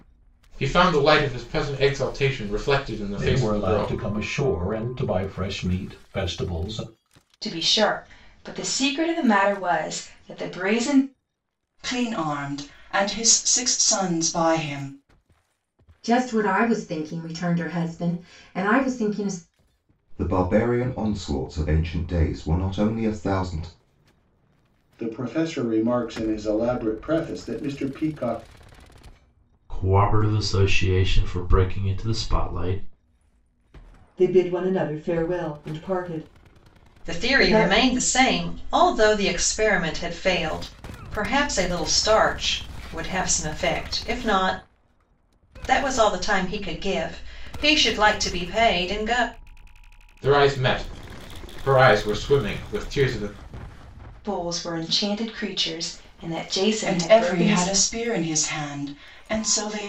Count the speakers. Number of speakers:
10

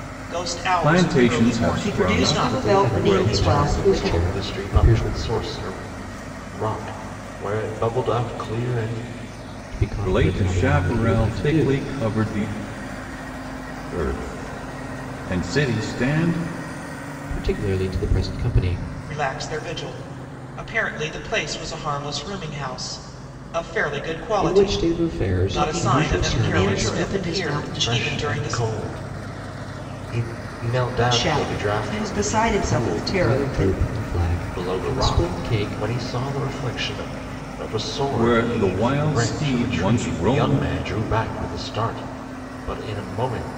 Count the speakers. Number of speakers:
5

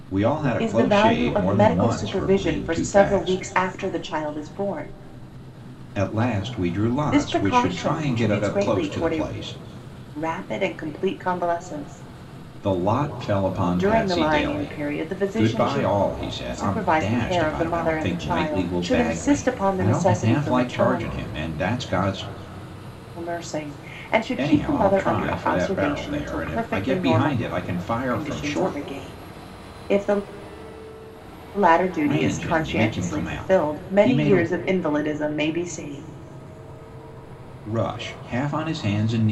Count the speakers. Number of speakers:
2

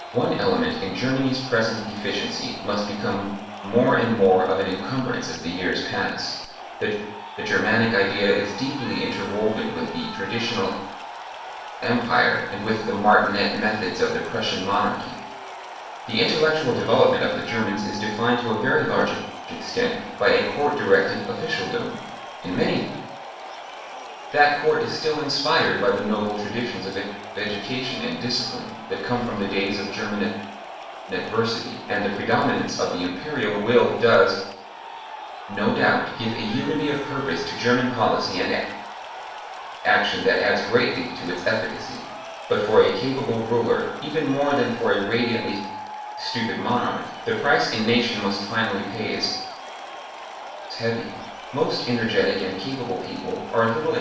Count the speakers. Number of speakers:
1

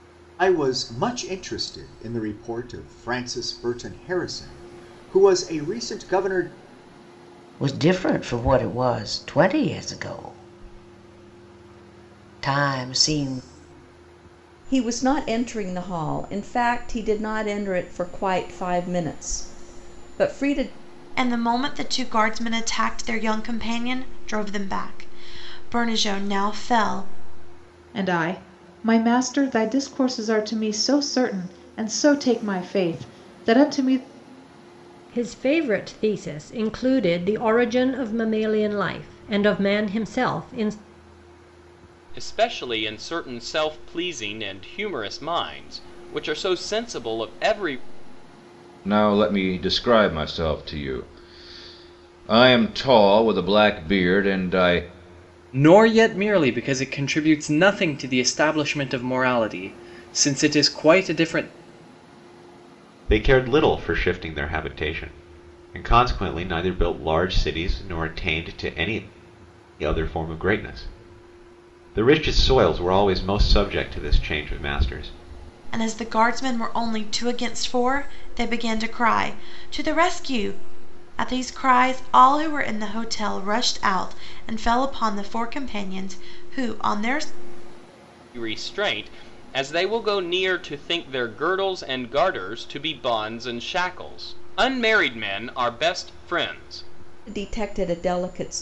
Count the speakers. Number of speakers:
10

